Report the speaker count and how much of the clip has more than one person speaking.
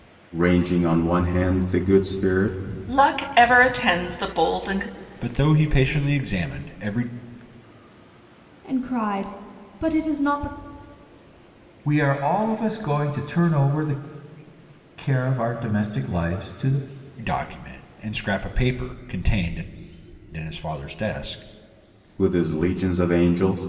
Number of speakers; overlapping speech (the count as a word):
five, no overlap